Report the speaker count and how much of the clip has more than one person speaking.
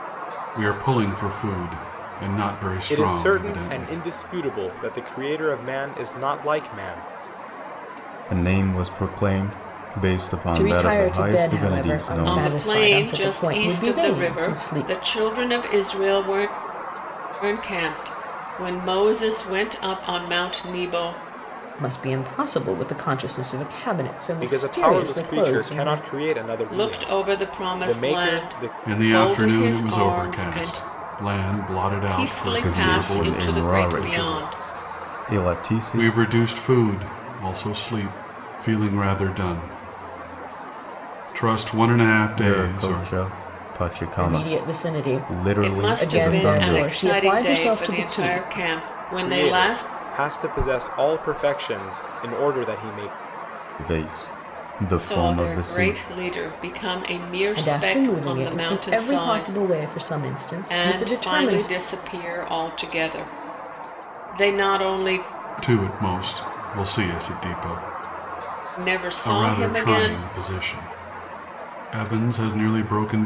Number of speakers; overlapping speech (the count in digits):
5, about 36%